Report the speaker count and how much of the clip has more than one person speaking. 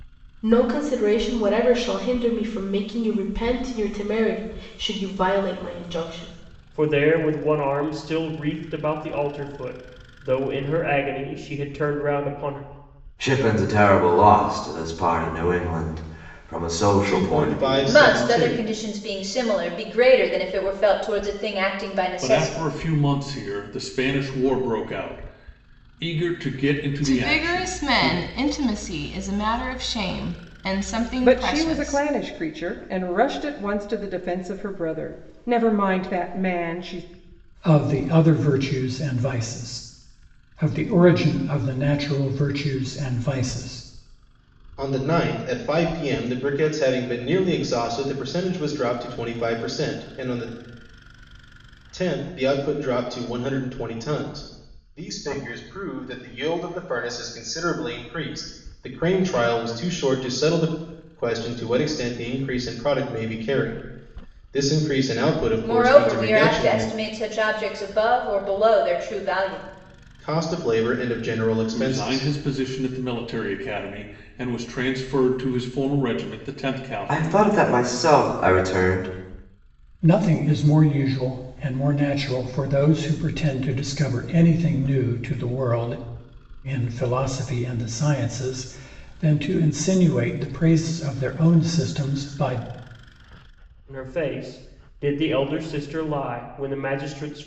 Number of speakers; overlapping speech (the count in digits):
9, about 7%